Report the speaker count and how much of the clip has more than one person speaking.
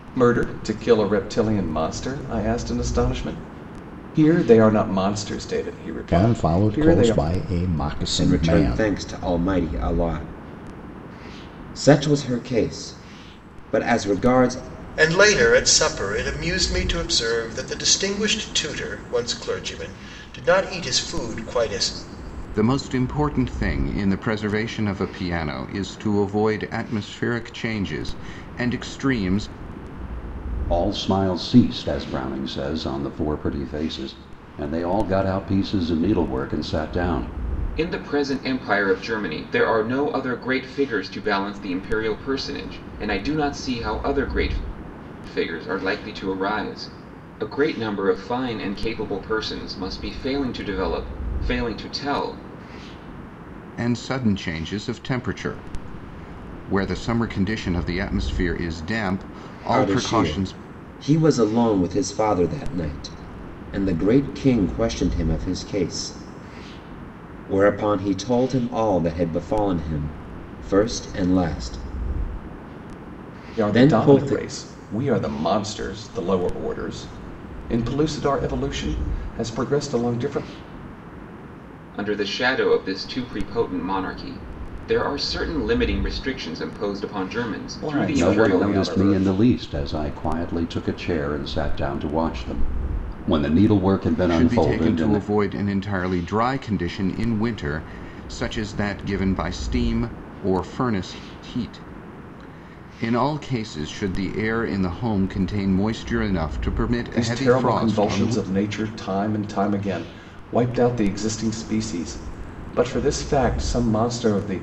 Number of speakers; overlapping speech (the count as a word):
seven, about 7%